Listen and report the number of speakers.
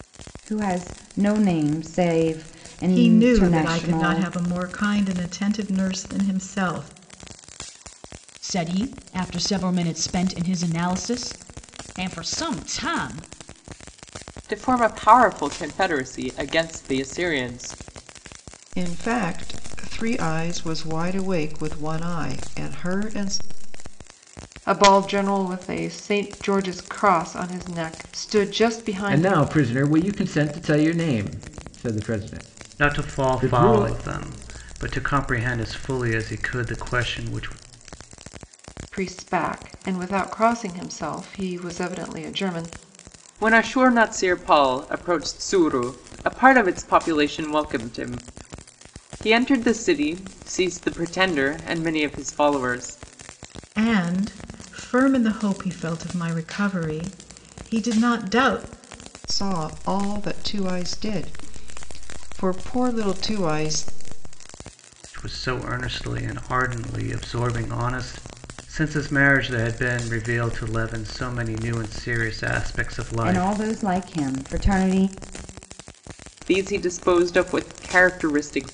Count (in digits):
8